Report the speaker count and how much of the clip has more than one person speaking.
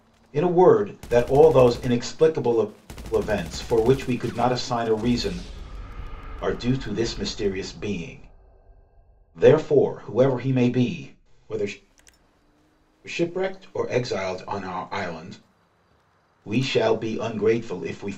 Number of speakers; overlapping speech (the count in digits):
1, no overlap